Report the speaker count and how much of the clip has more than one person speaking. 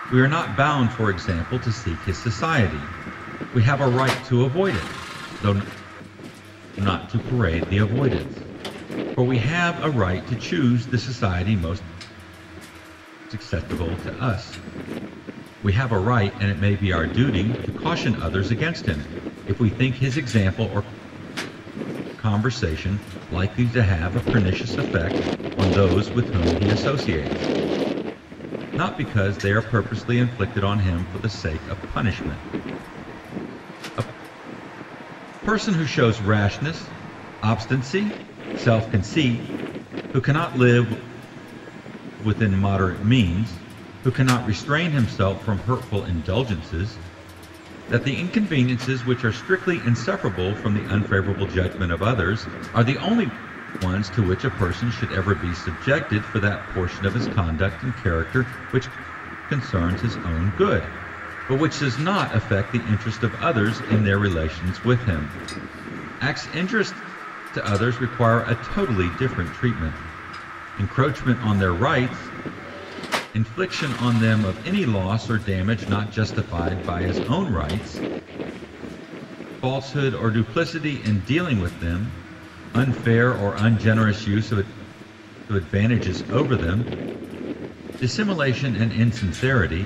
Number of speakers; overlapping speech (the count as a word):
one, no overlap